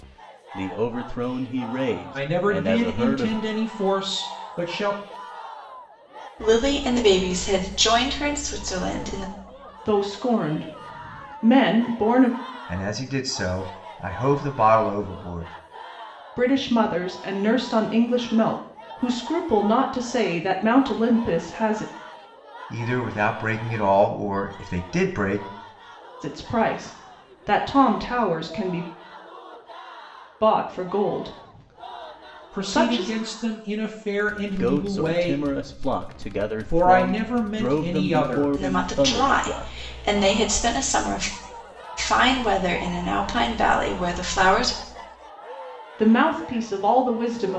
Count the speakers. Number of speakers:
5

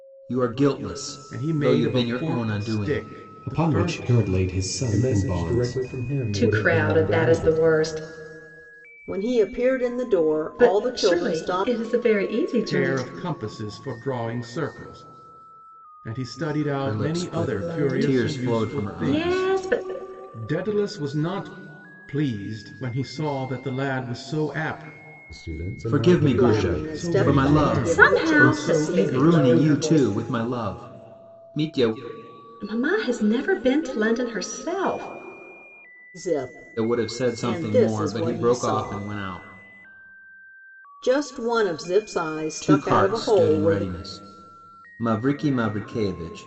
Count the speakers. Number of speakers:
6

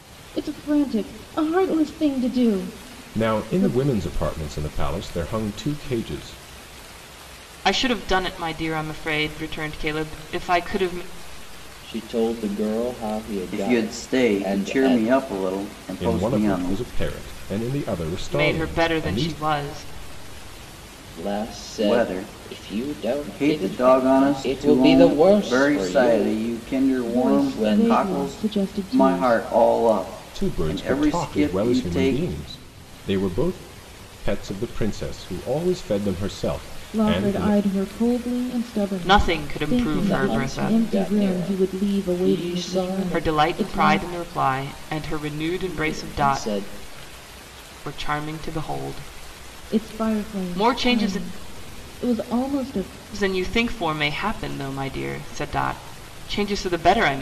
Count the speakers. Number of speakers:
5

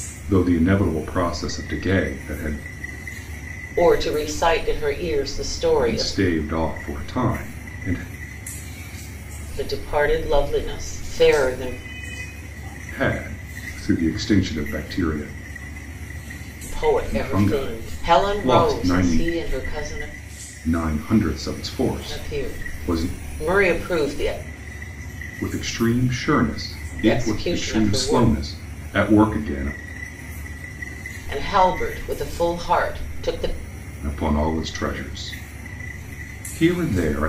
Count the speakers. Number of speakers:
2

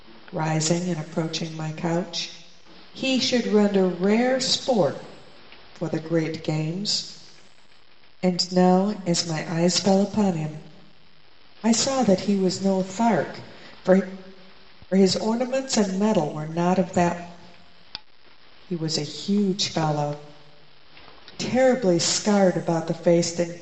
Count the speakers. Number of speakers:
1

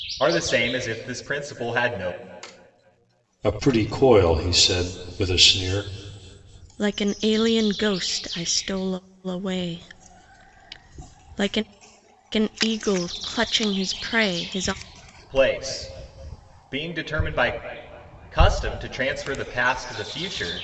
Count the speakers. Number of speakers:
3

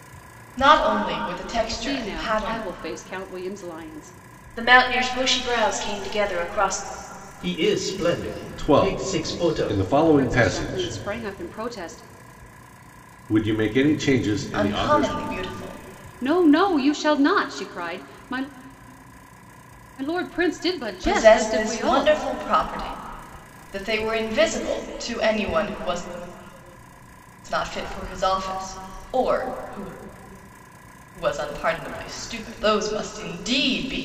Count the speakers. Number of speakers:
5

